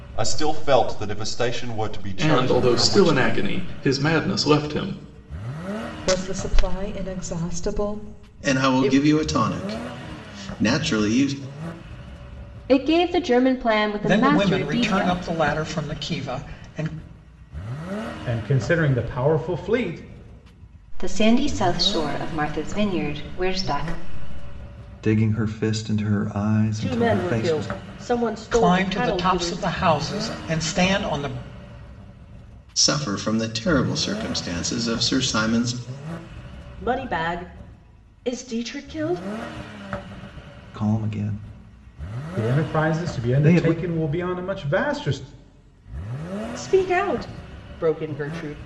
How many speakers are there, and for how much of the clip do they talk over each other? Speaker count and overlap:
10, about 14%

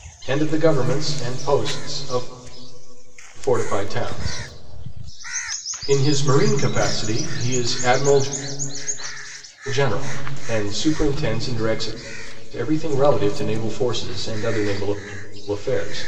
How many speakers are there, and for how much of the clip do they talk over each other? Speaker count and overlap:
1, no overlap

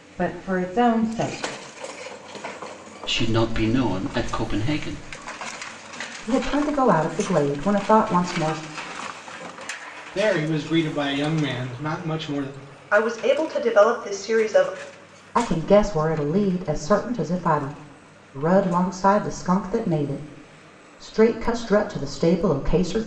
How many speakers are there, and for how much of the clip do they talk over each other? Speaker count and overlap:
5, no overlap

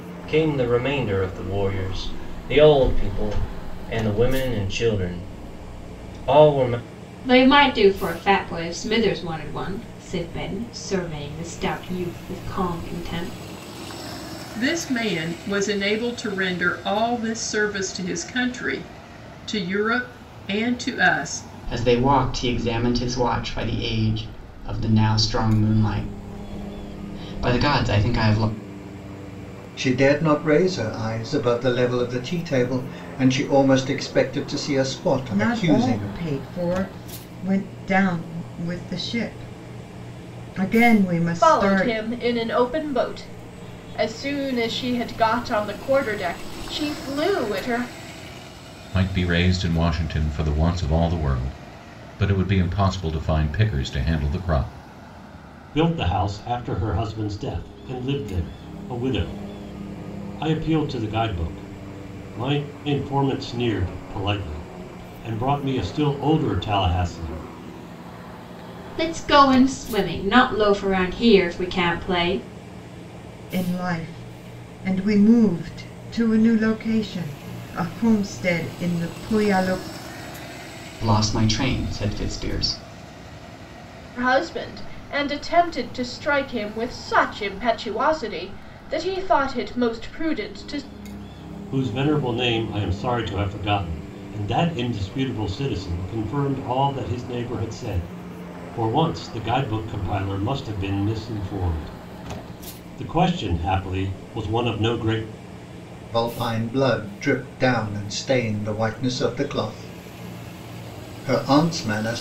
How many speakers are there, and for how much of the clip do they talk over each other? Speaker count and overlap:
9, about 1%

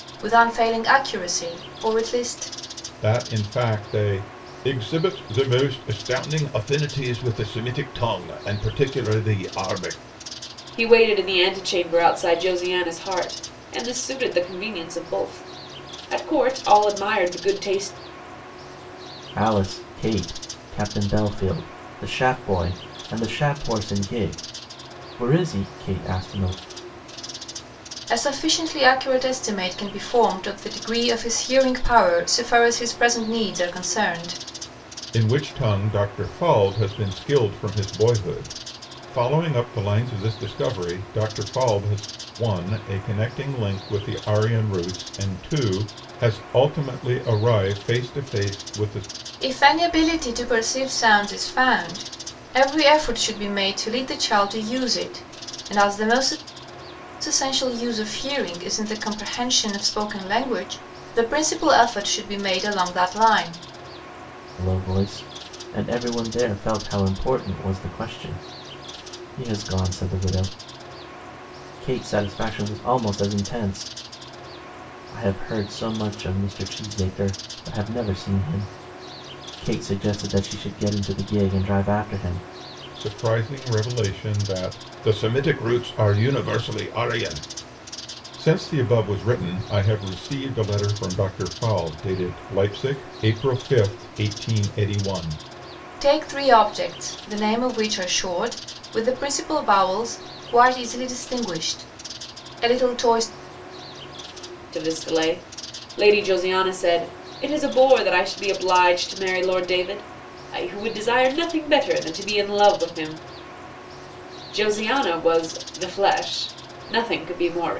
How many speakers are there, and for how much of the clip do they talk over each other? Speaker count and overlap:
4, no overlap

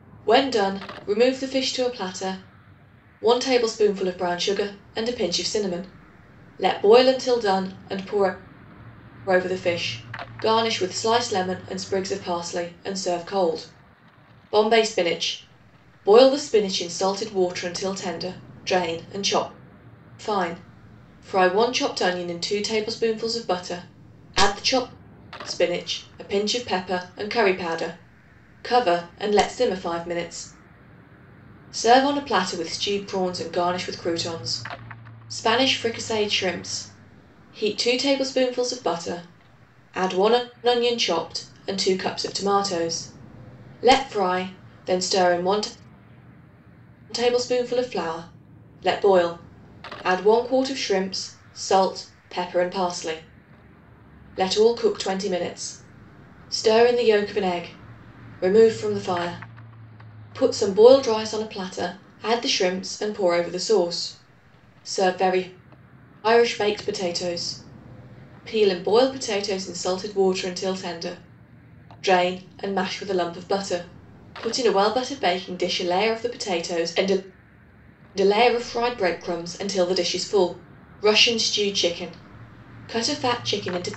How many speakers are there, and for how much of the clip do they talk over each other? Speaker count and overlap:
1, no overlap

